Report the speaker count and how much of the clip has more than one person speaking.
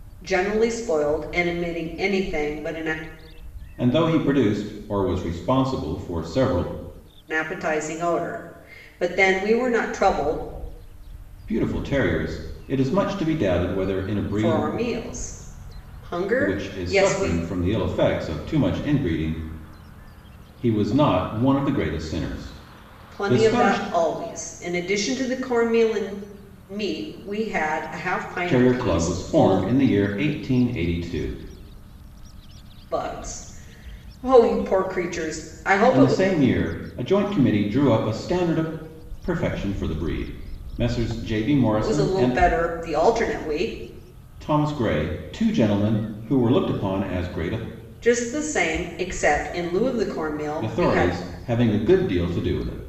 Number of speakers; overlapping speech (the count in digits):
2, about 10%